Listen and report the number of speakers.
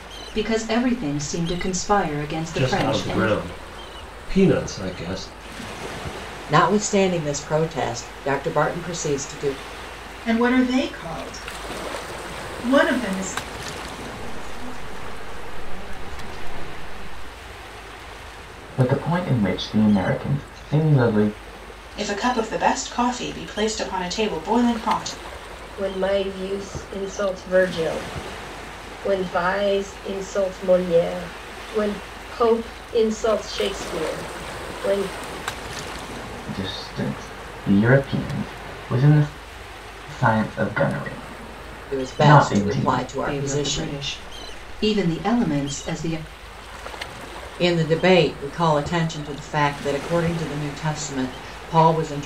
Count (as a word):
eight